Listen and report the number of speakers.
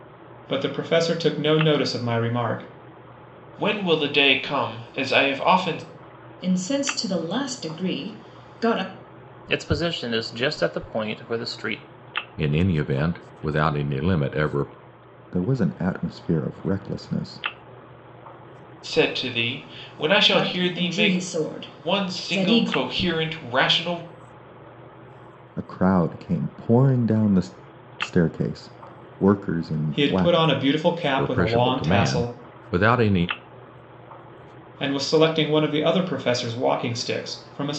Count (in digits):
6